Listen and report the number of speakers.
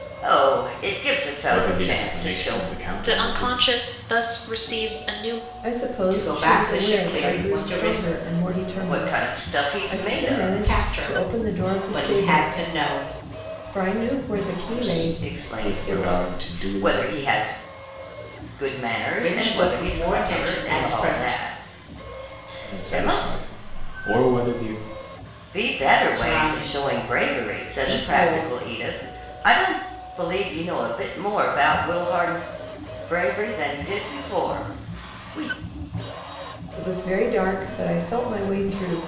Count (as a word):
five